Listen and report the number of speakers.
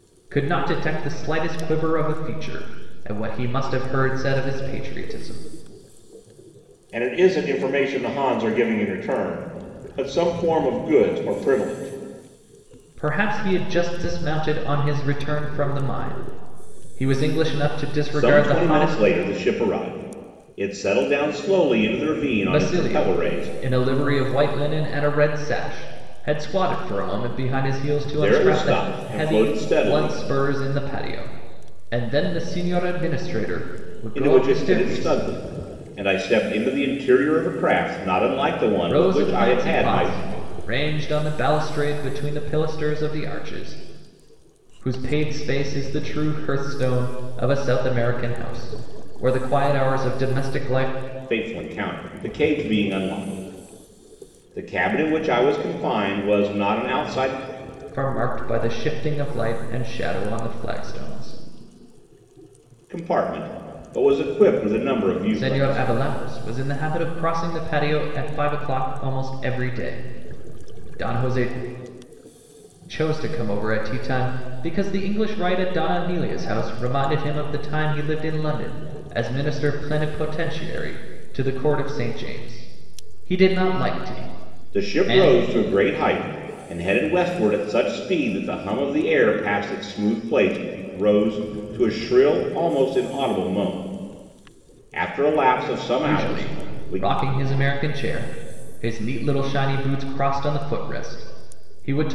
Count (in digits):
2